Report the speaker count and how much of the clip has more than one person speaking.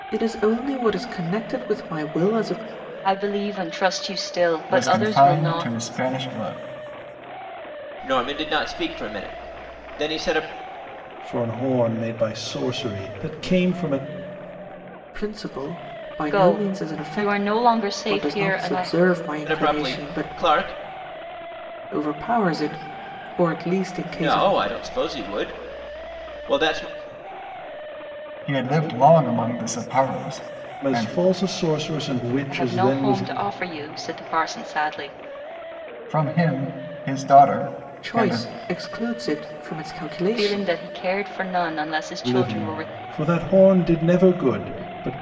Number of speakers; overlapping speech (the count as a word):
five, about 16%